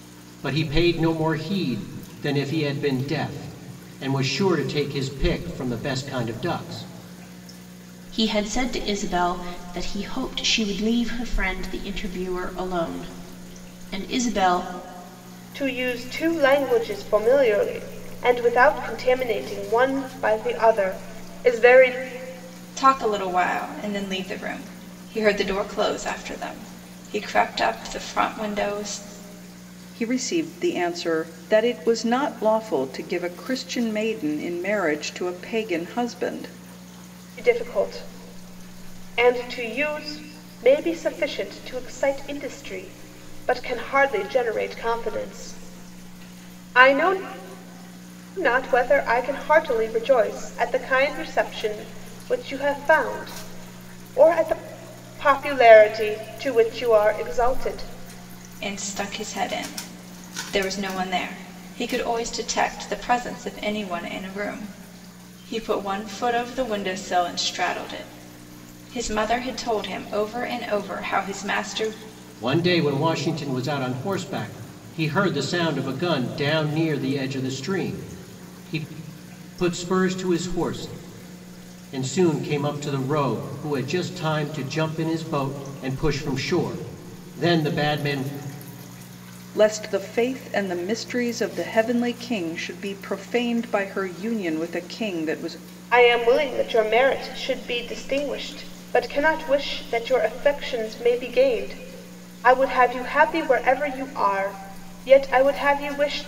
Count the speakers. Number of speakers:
5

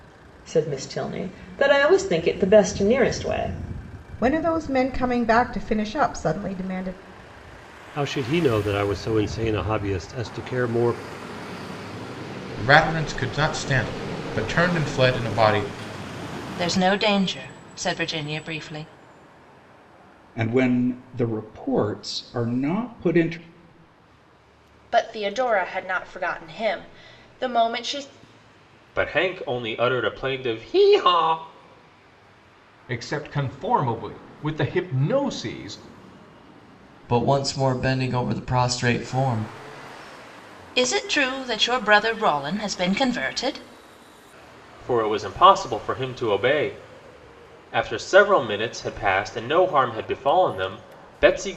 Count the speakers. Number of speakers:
10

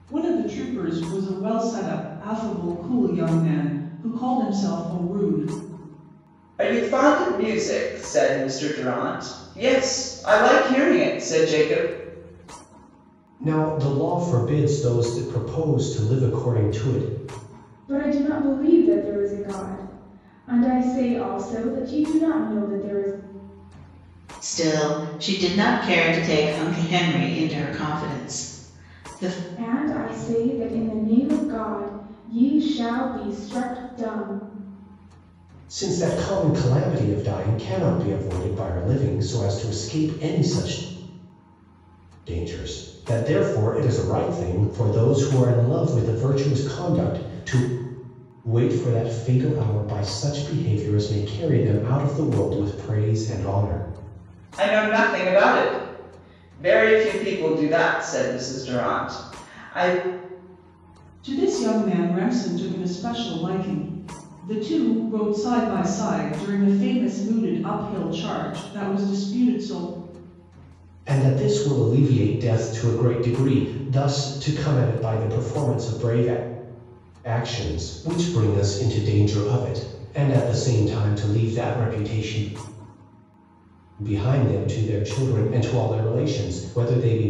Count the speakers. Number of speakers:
5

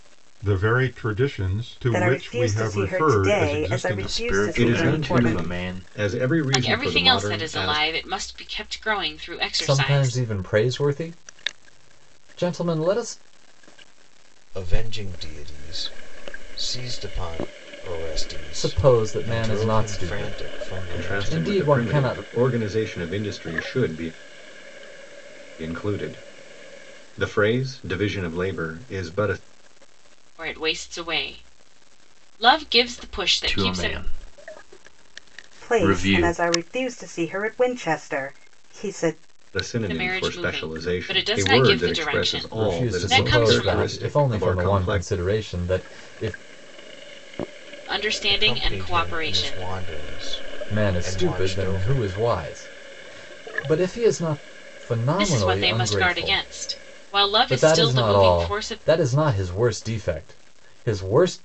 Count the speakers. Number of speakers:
7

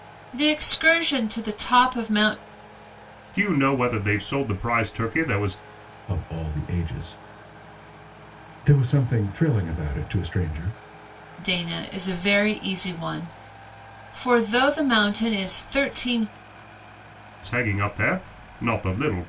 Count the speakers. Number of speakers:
3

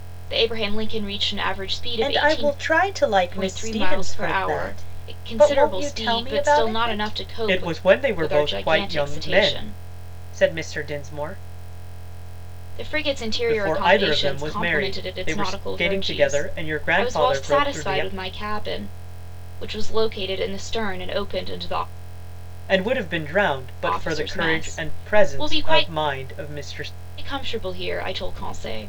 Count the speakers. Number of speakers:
2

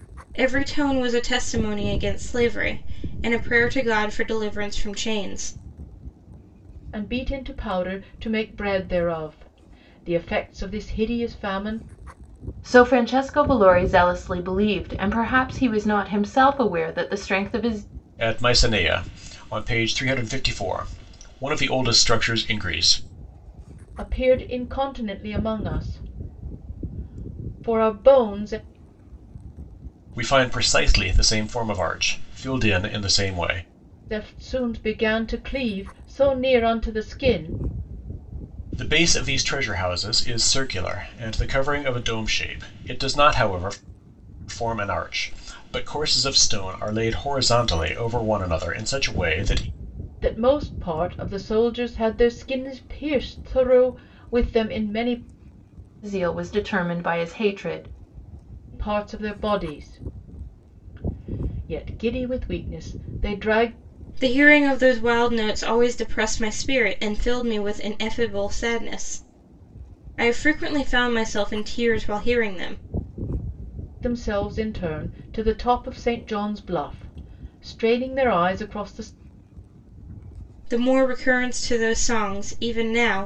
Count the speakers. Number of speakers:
4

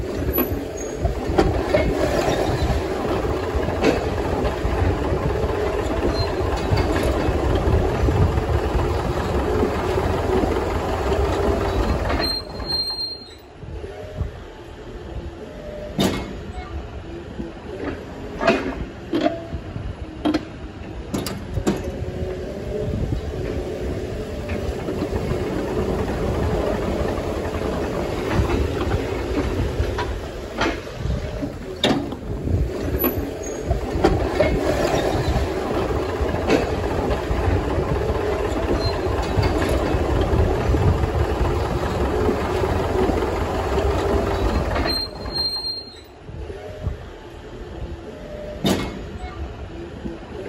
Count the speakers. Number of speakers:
0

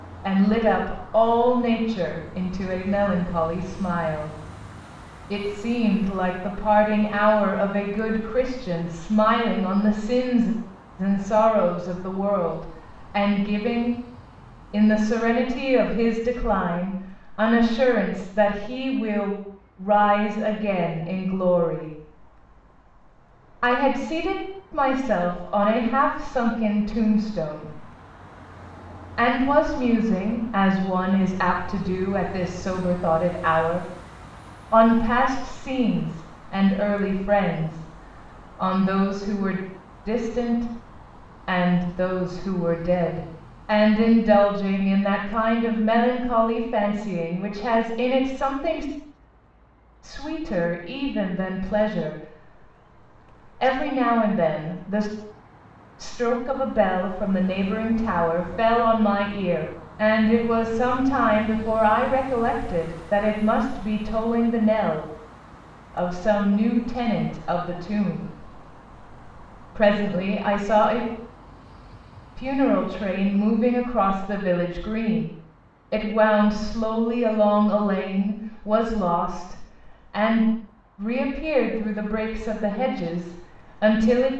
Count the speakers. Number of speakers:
1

